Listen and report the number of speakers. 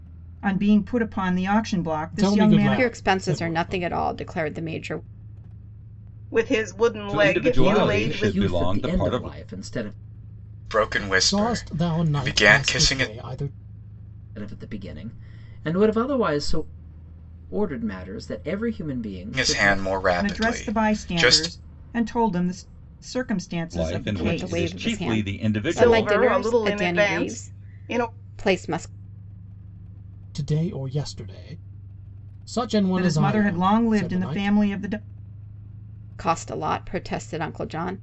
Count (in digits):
7